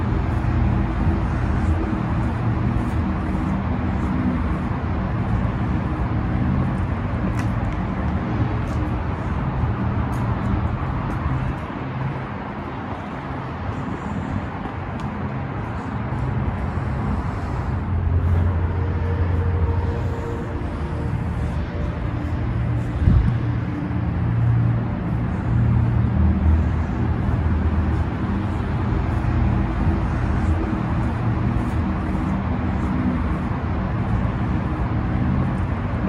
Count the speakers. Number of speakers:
zero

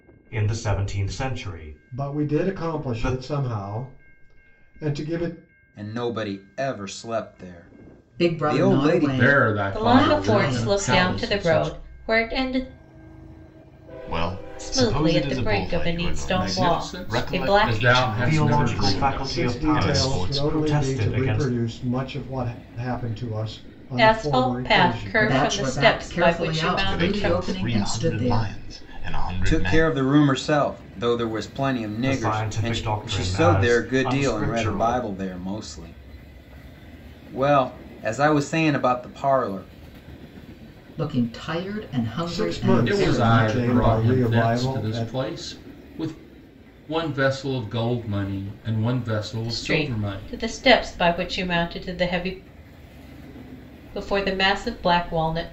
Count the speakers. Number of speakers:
seven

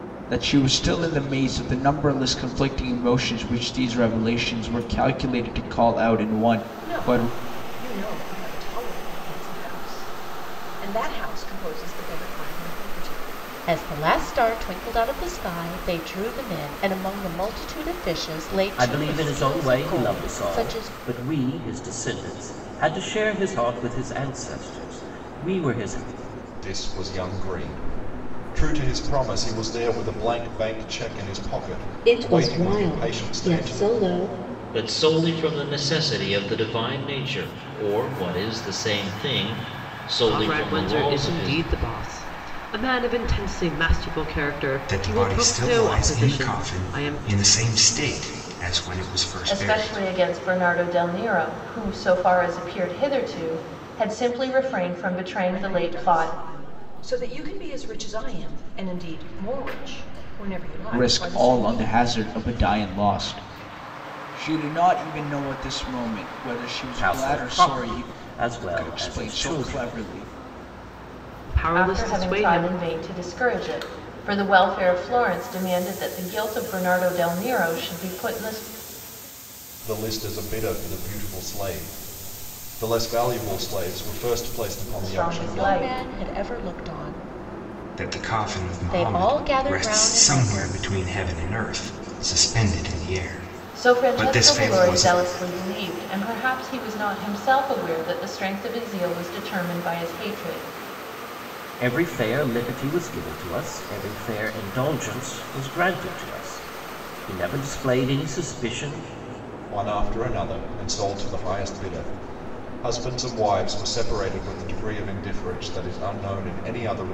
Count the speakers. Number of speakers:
ten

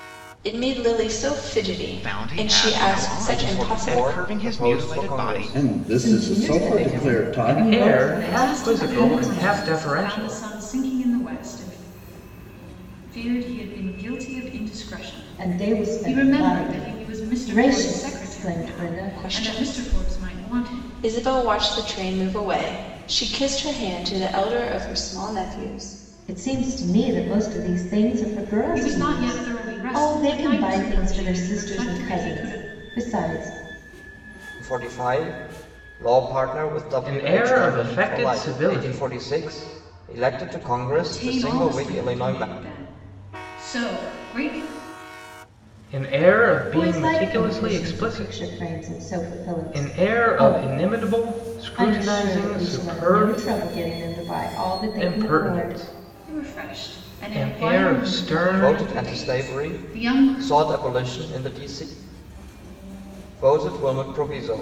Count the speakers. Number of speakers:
seven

